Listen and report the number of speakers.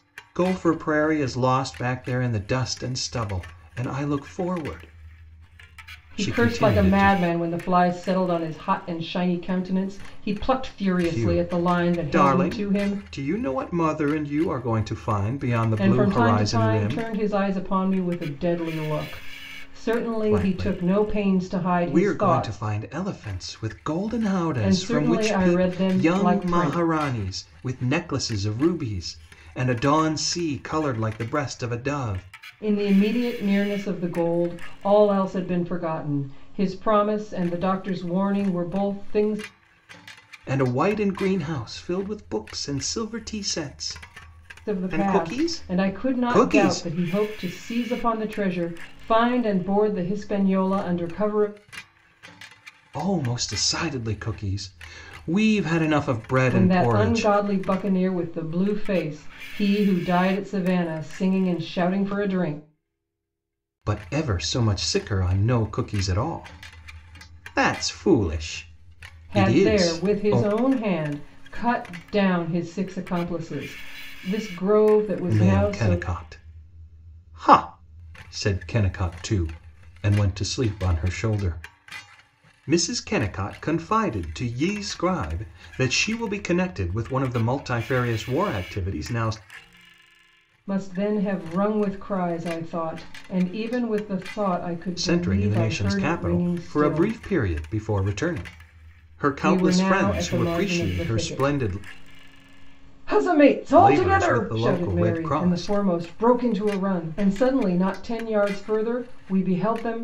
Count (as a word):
two